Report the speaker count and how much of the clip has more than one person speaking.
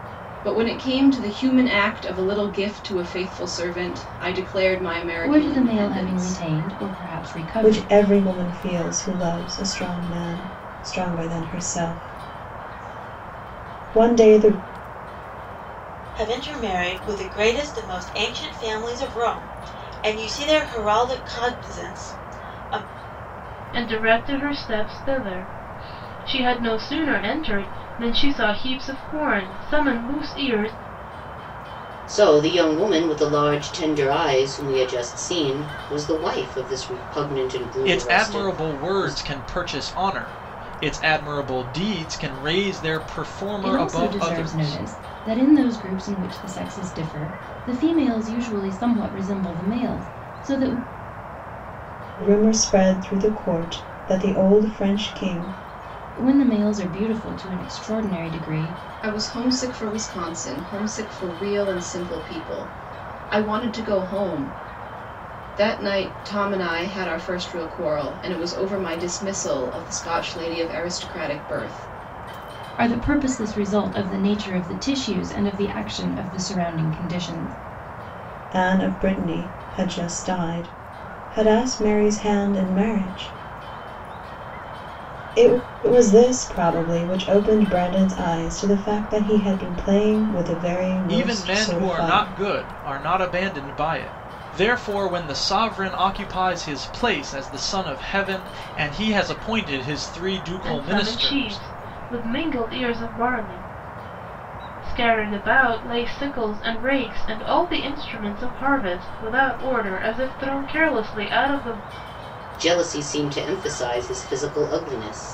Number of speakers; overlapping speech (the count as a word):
seven, about 6%